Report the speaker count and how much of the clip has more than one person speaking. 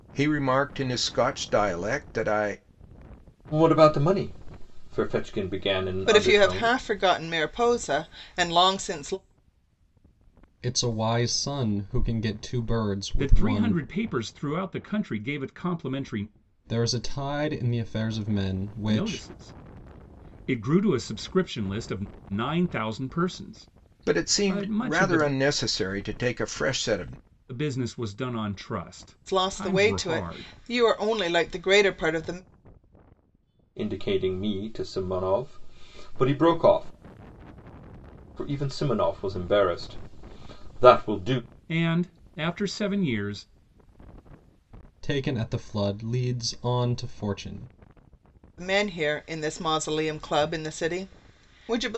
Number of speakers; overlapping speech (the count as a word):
five, about 8%